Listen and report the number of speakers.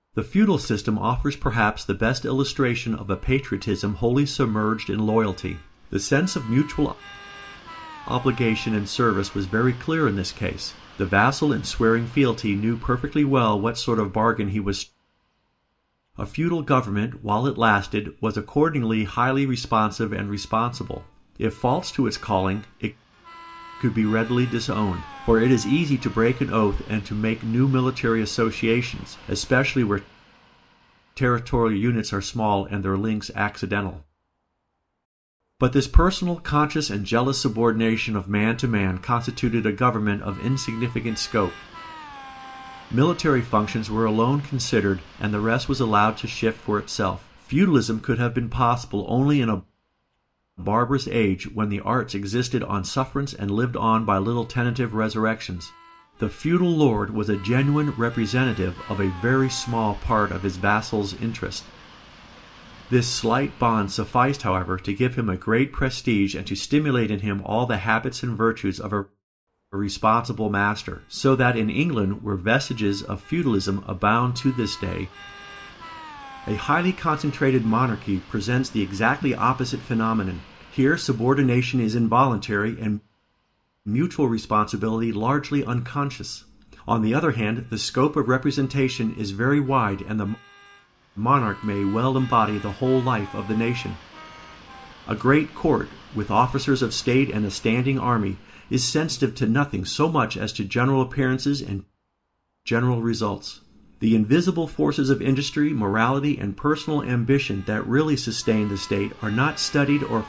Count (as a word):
one